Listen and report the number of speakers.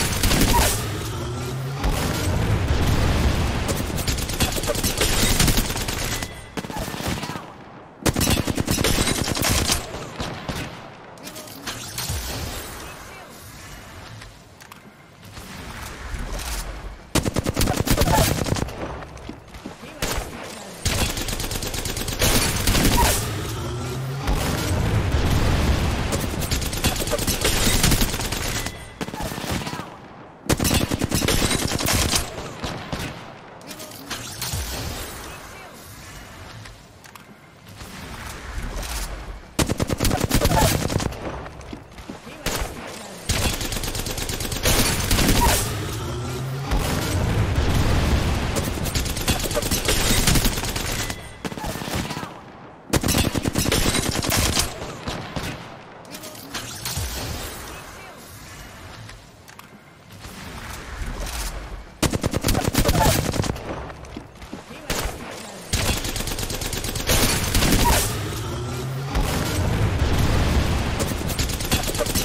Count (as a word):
zero